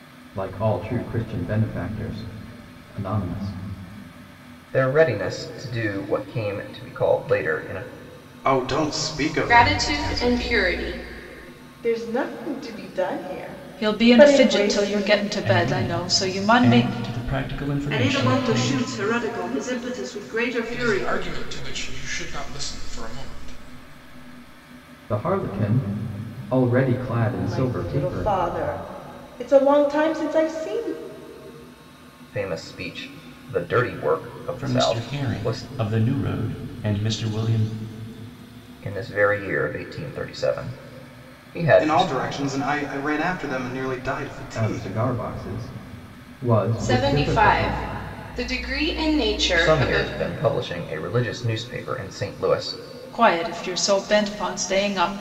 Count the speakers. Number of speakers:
nine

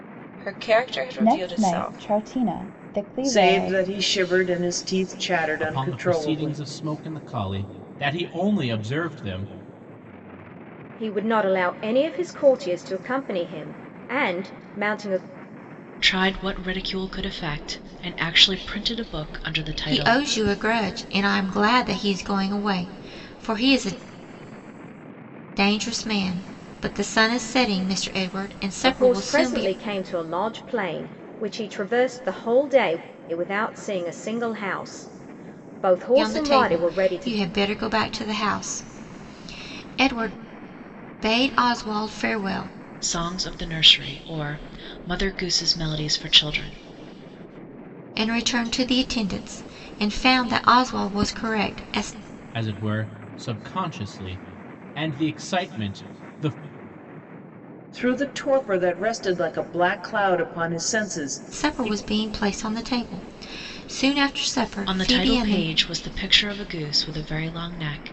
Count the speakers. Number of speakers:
seven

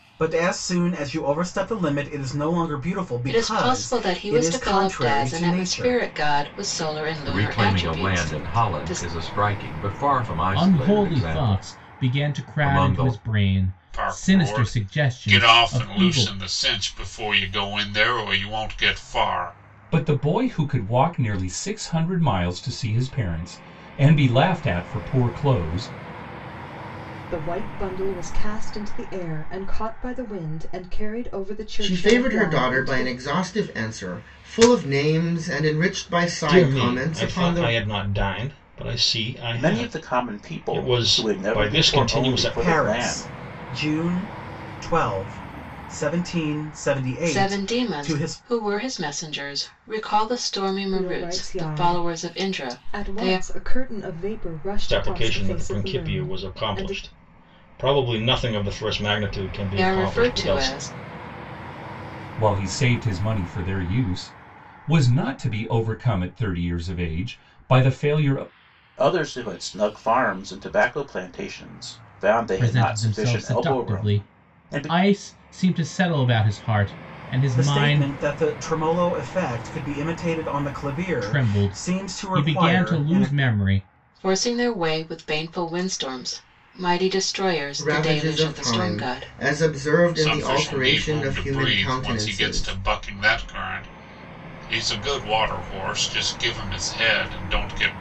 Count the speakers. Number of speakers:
ten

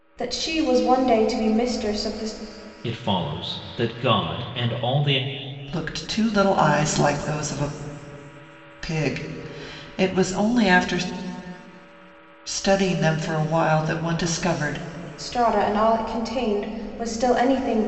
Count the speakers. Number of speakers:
three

